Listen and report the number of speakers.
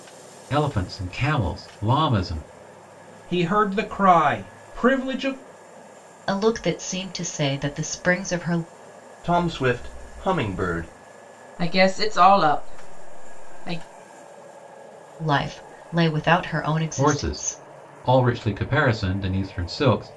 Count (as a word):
five